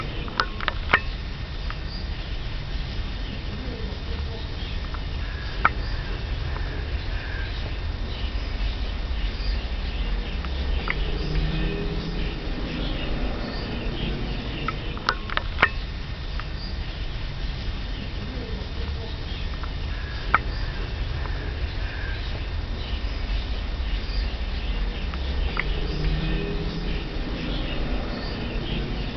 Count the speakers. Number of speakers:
zero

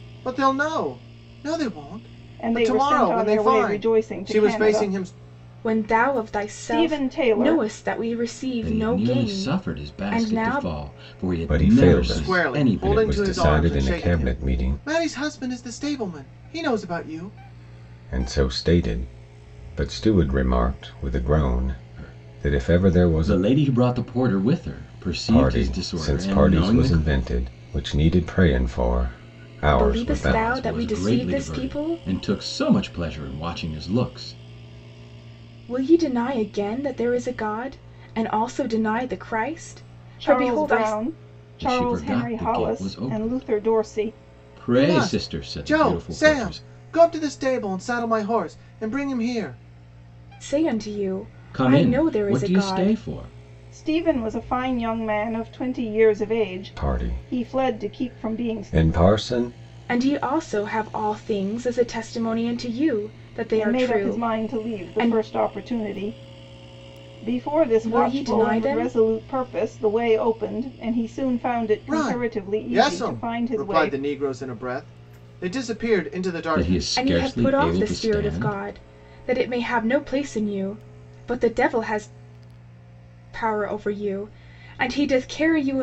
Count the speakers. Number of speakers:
five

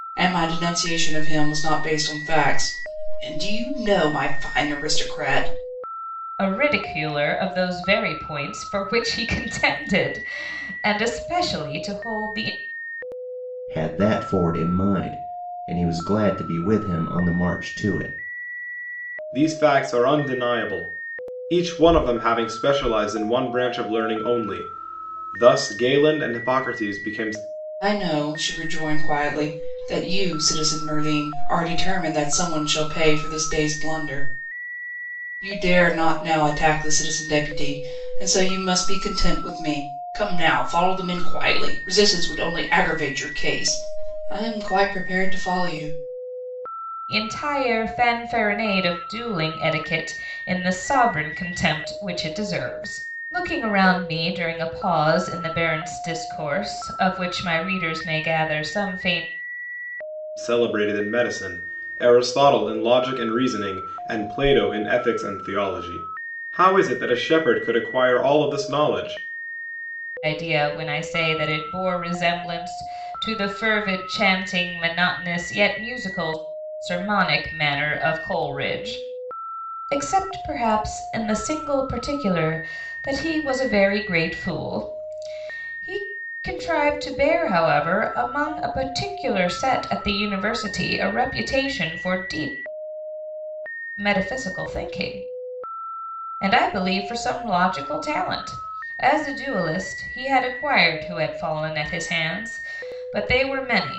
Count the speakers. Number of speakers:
four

